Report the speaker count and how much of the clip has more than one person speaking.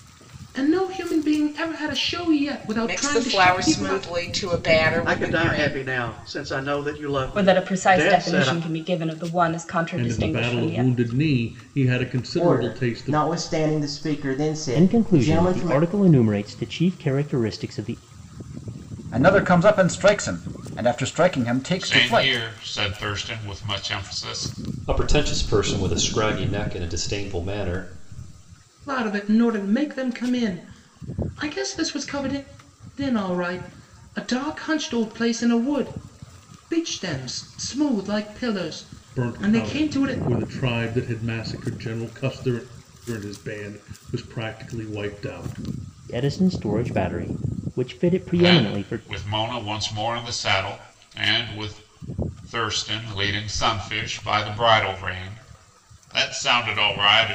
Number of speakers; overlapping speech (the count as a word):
ten, about 15%